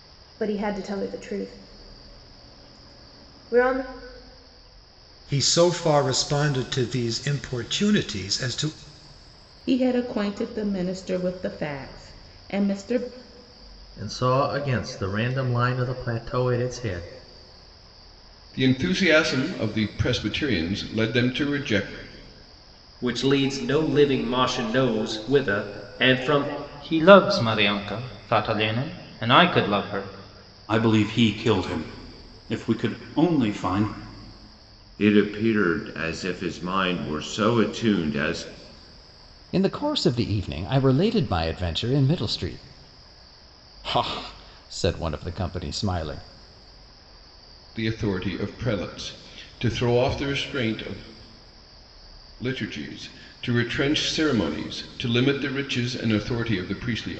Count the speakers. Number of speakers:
10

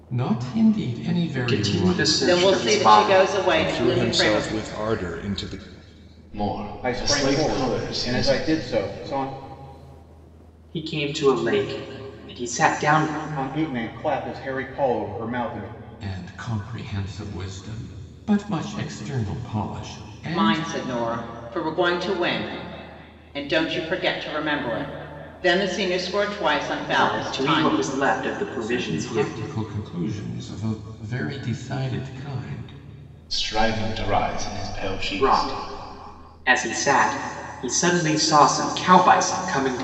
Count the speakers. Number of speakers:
6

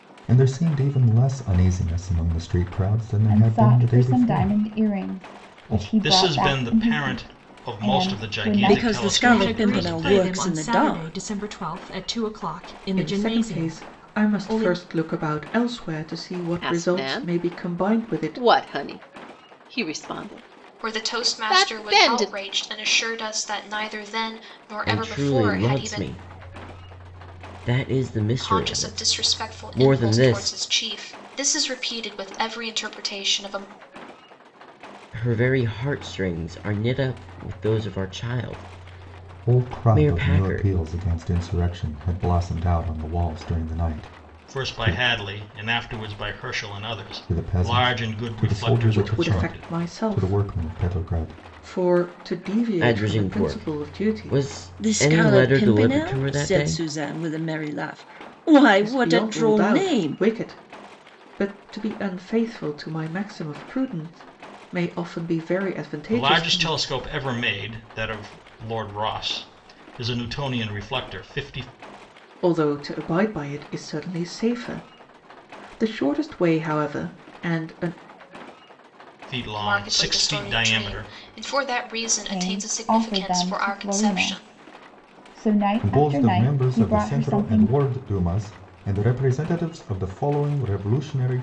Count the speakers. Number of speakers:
9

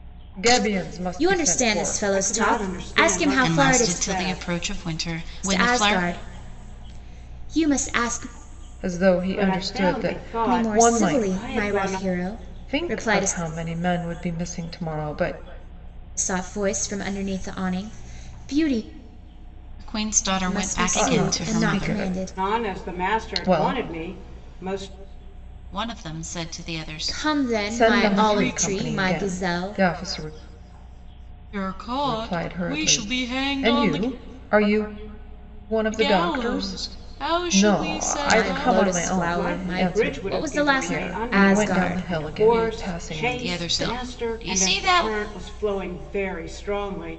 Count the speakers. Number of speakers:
4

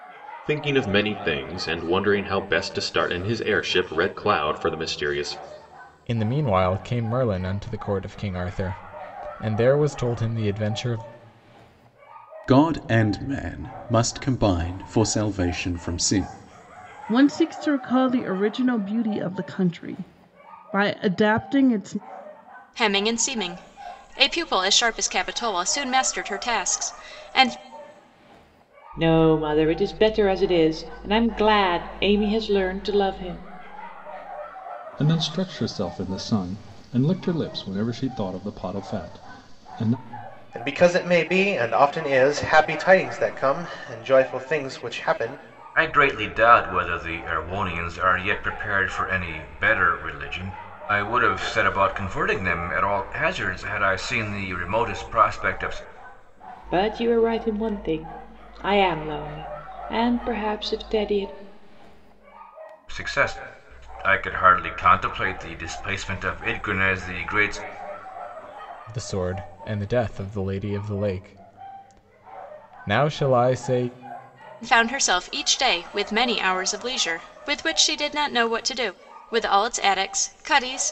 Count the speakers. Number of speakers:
9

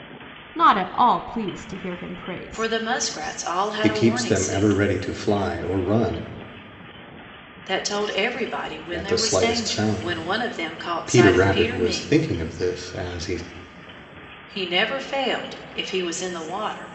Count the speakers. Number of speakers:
3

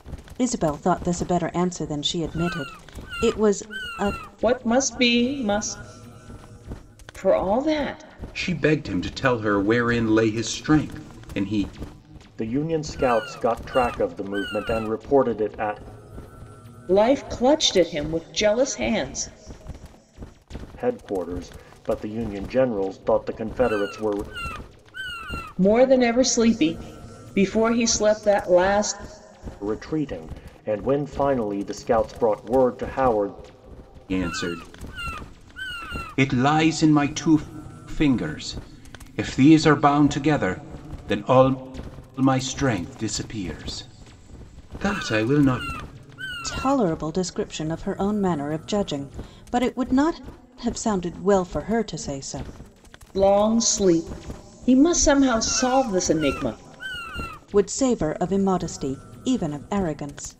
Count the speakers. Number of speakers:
4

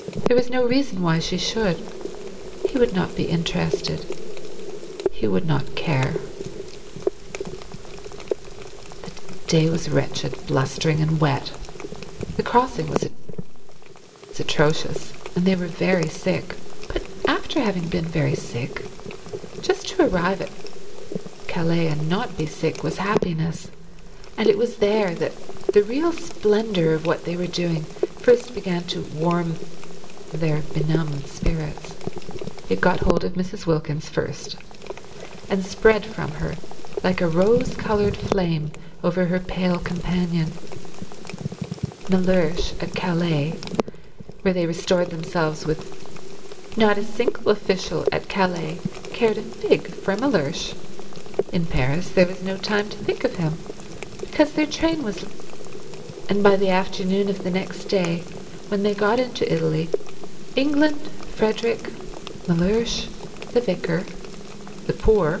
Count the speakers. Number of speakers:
1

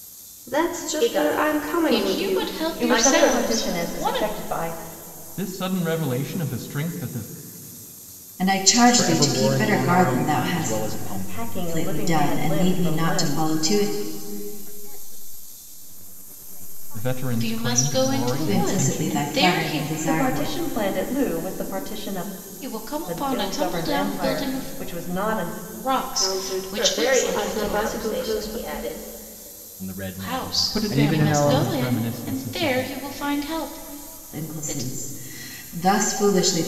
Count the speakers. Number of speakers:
8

